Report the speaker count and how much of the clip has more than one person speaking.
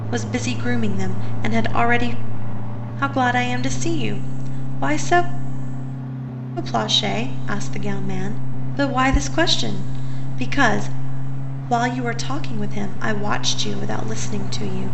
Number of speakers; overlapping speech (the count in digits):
1, no overlap